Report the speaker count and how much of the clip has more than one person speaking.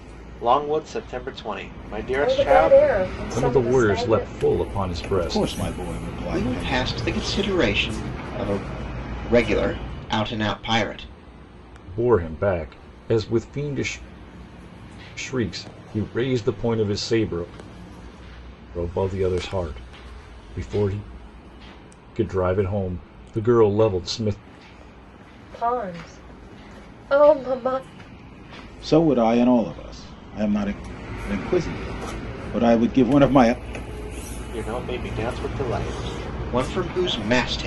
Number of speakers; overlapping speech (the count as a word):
five, about 9%